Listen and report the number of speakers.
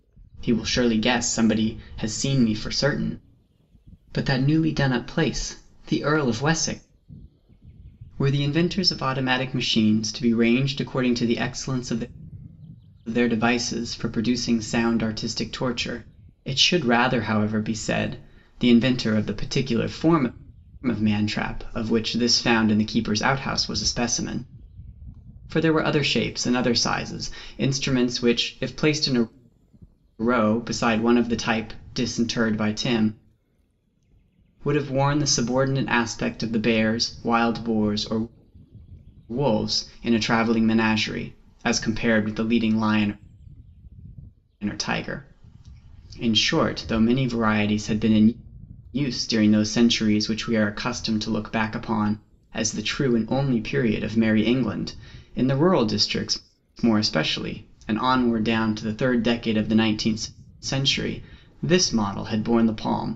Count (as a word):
one